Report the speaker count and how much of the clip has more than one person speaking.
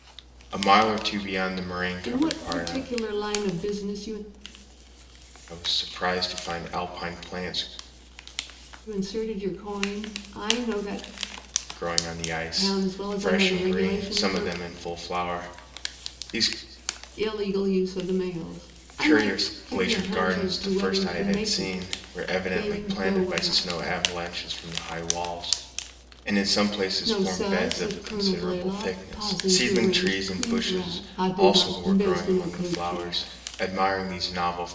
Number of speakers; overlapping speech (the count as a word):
two, about 37%